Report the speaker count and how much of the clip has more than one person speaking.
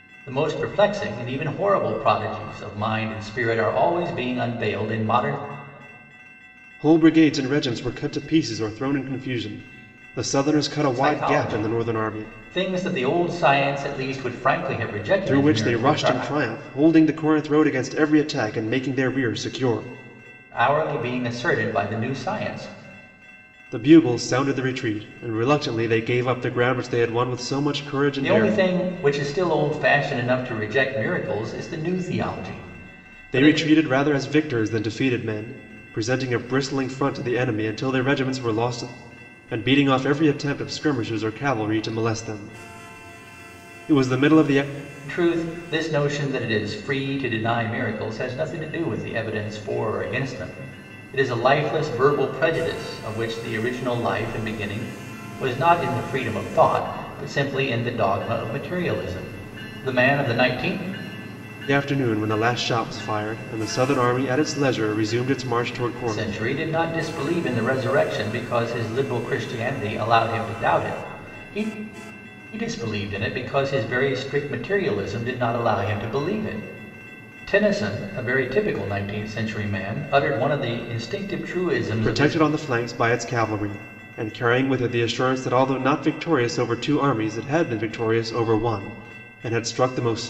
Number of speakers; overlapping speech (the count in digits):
2, about 5%